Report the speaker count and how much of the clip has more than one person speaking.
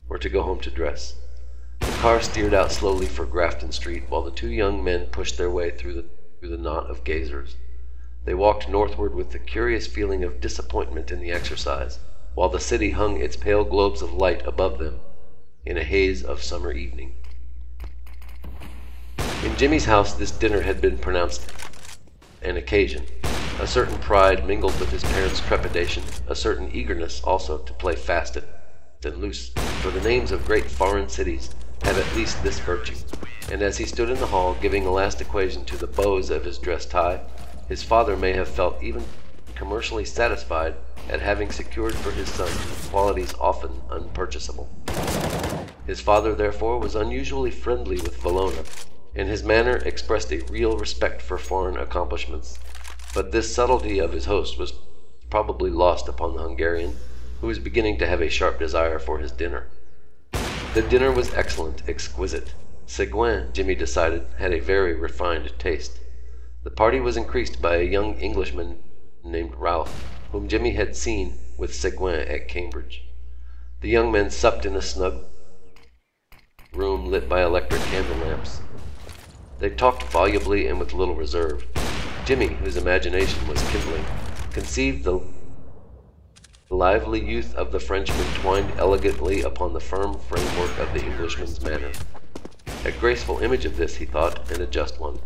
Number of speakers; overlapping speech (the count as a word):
one, no overlap